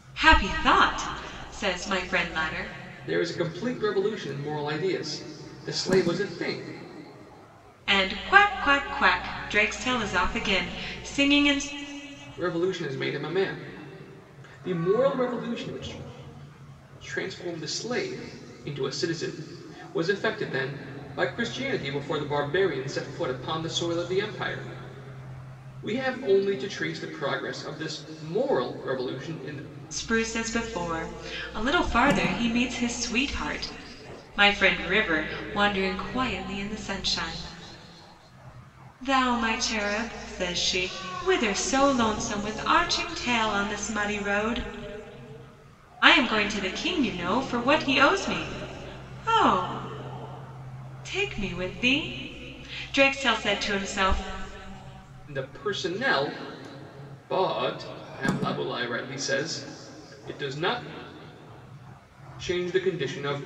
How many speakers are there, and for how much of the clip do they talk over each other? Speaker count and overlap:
two, no overlap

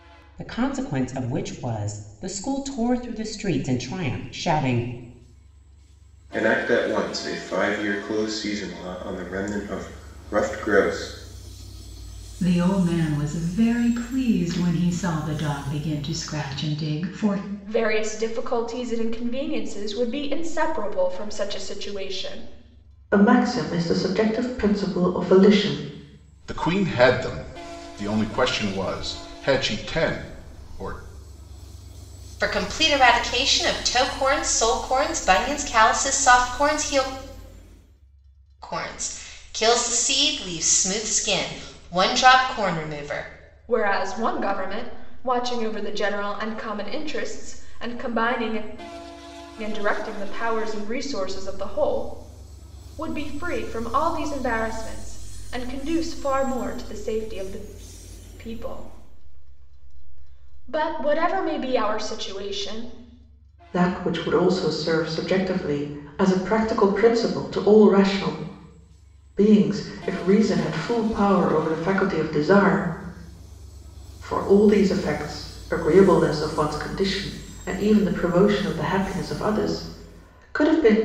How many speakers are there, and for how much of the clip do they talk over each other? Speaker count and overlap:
seven, no overlap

